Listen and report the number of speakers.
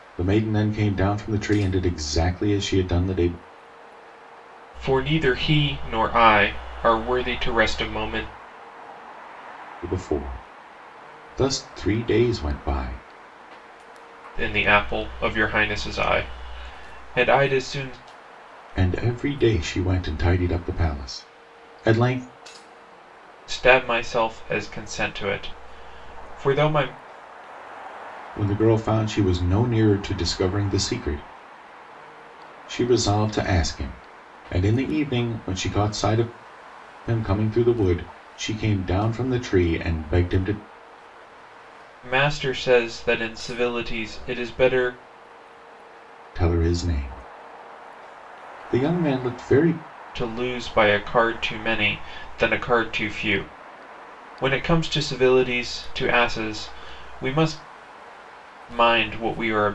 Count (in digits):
2